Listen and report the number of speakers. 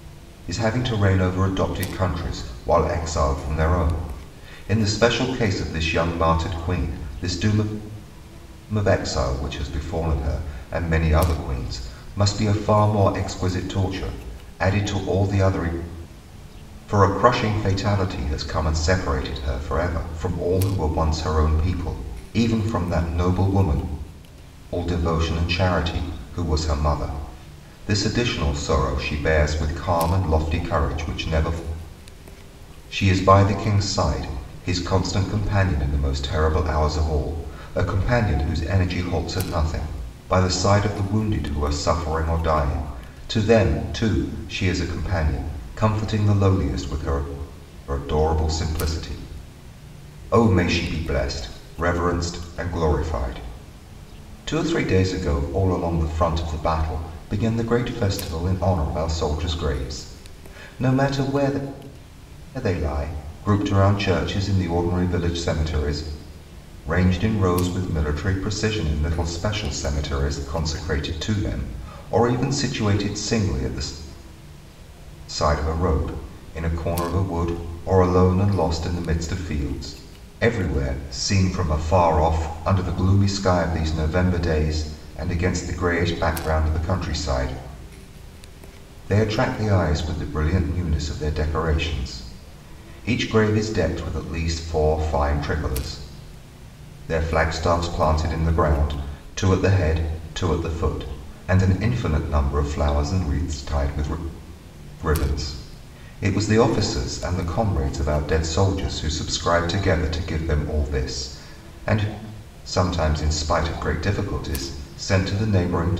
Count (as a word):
one